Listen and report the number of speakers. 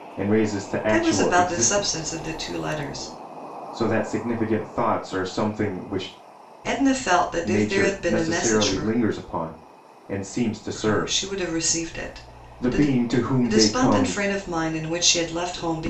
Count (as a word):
two